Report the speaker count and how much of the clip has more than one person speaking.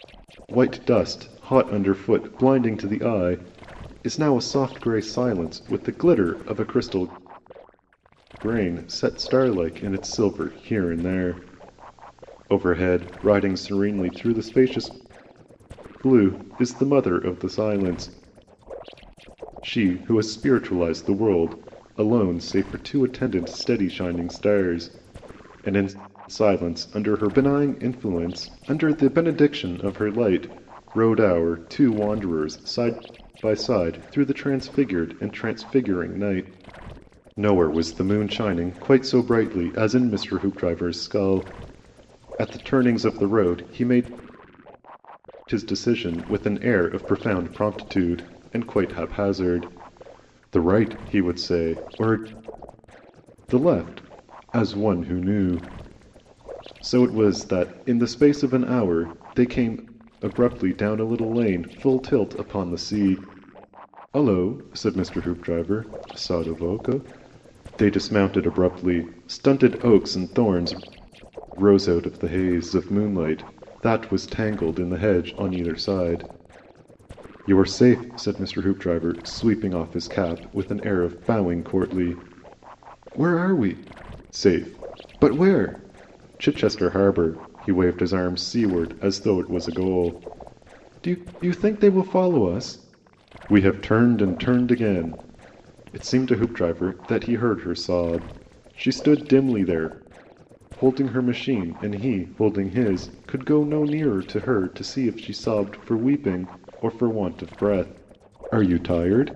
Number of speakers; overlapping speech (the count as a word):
one, no overlap